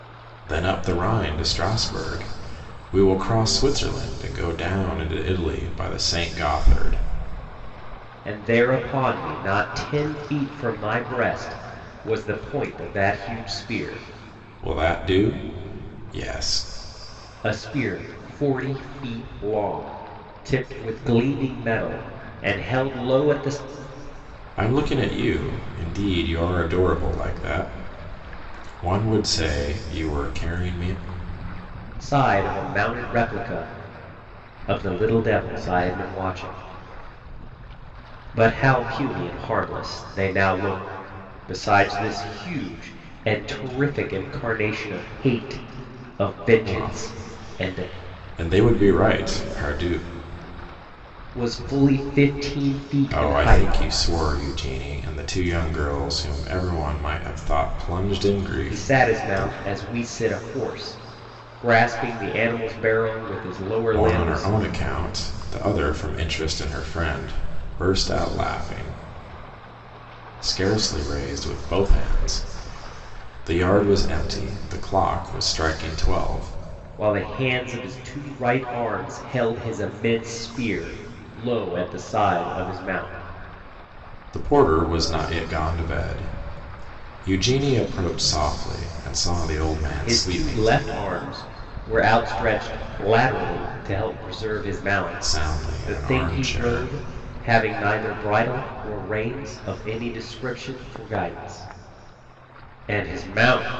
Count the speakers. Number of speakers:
2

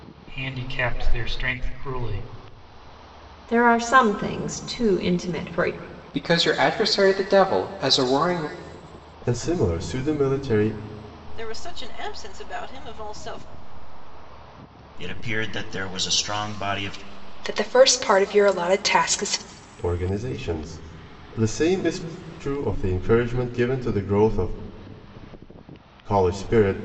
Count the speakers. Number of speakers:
7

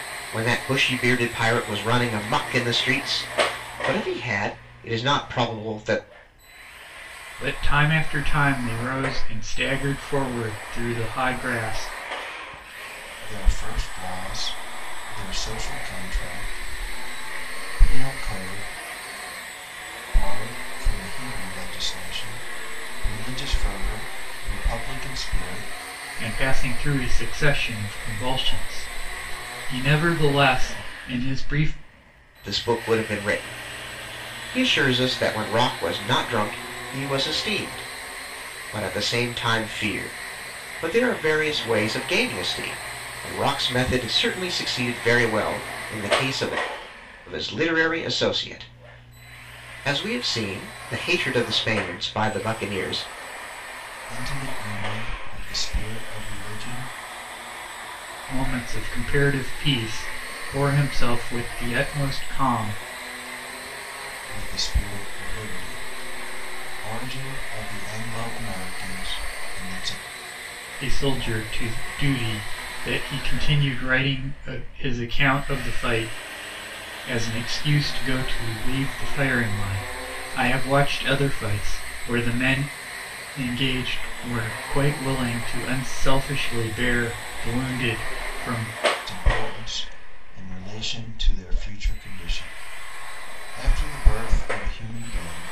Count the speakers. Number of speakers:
3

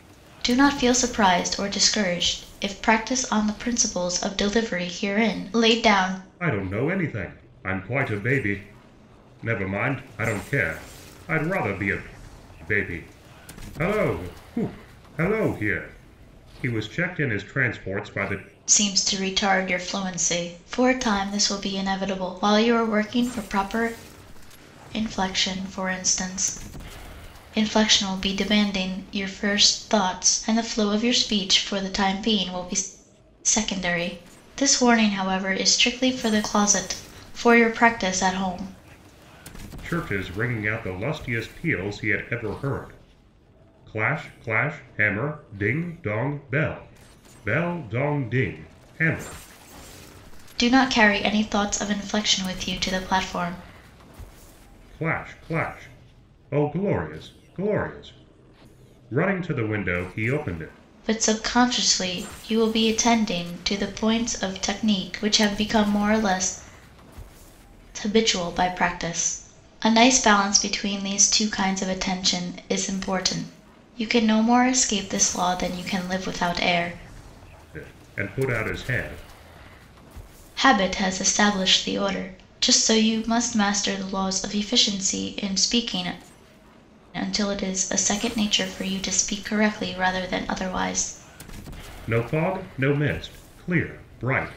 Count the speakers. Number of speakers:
2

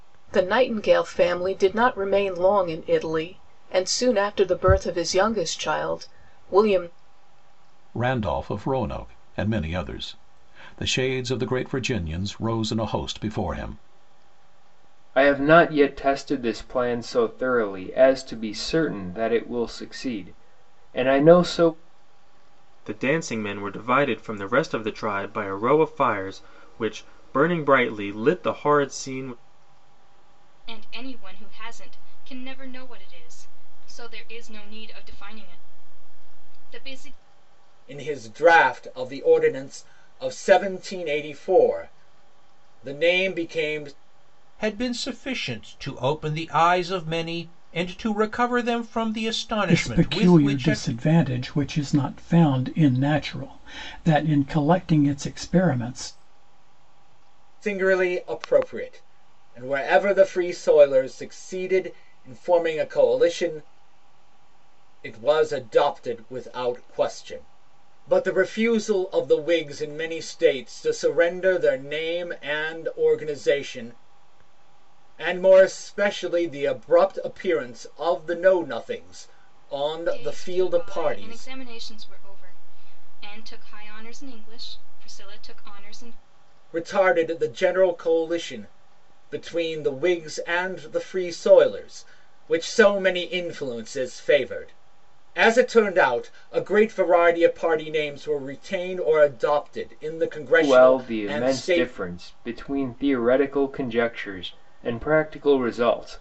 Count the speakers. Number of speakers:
8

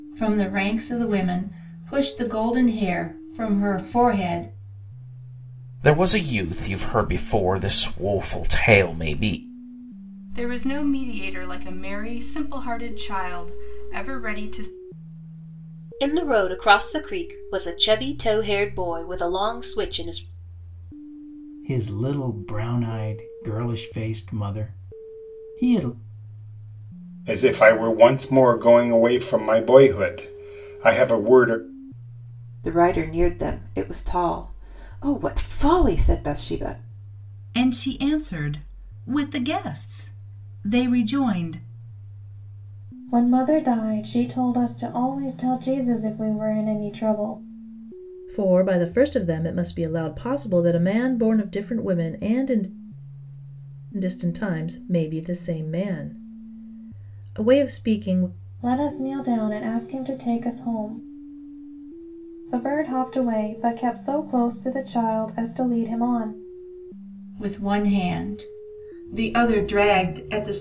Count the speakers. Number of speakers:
10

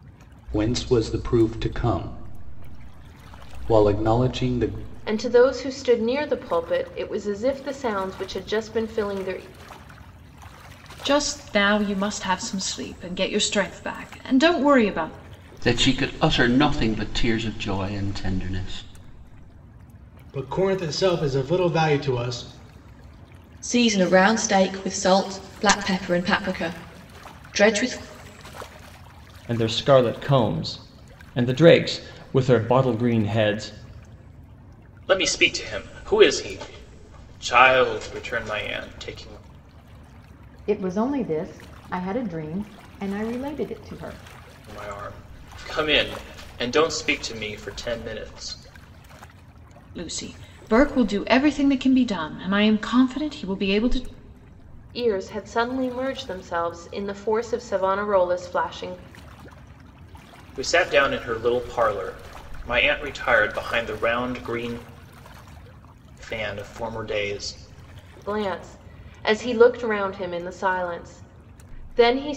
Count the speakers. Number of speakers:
9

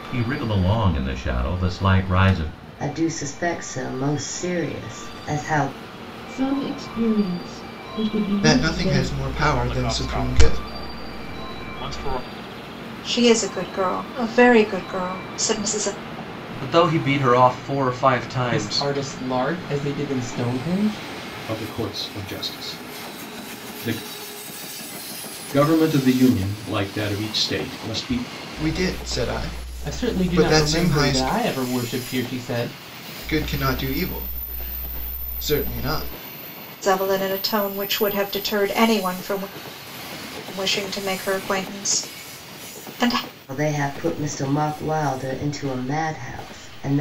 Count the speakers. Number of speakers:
9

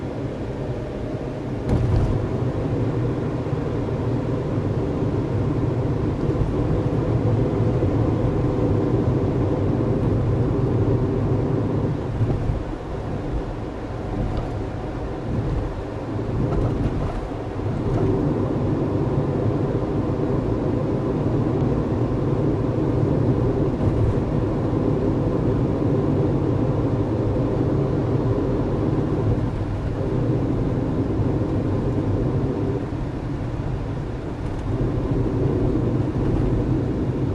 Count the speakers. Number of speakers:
0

